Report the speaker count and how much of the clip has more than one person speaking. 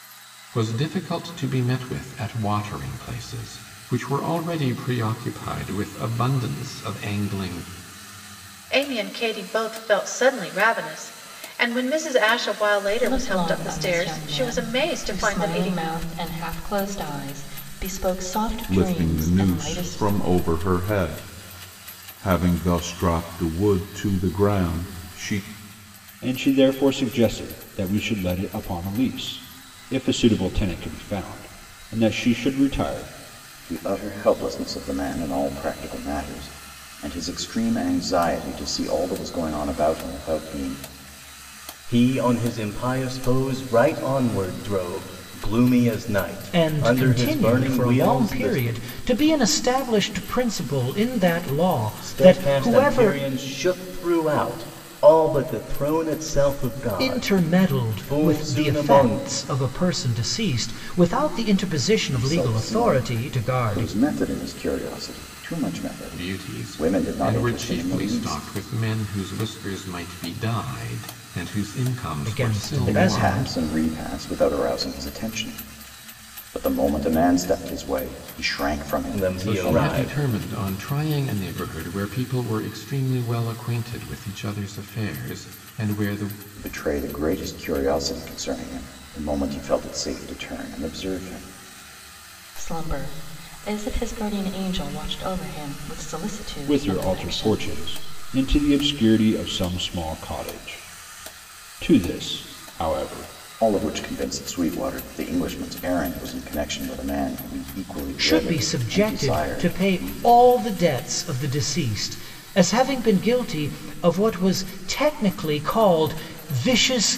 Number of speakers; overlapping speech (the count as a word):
eight, about 17%